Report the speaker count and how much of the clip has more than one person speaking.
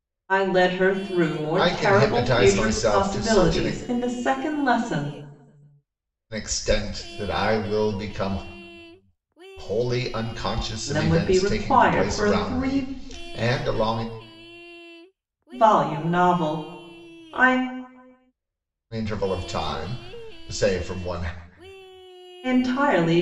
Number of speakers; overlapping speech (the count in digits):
2, about 18%